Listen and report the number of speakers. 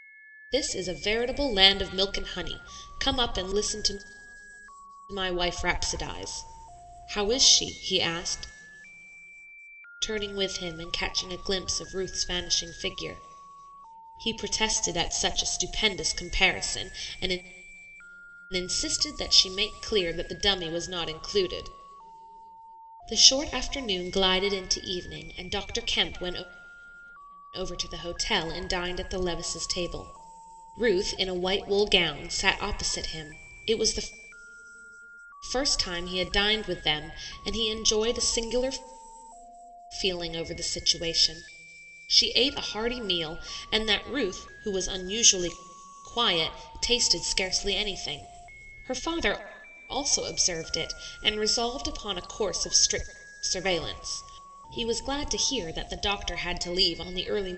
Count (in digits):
1